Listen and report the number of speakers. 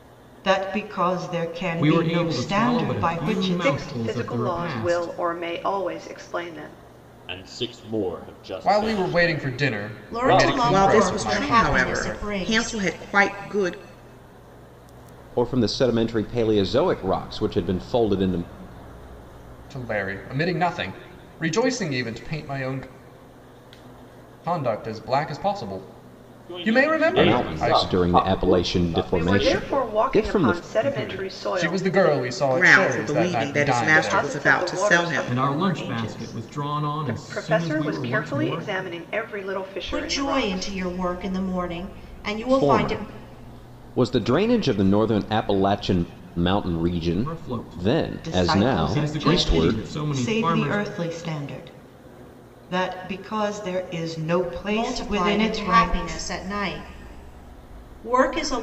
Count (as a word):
eight